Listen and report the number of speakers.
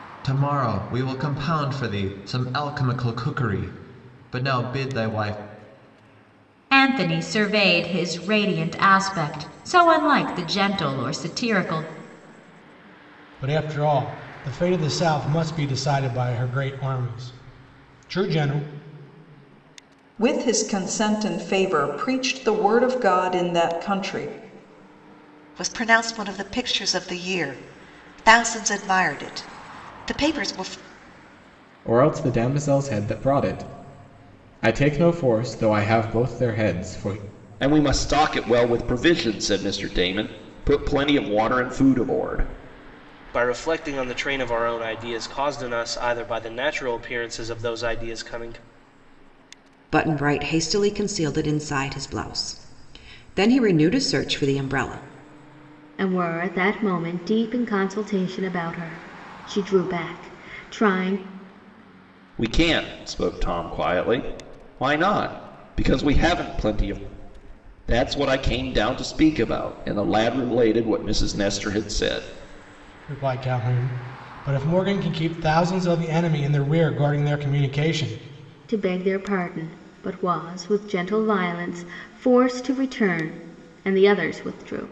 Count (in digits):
10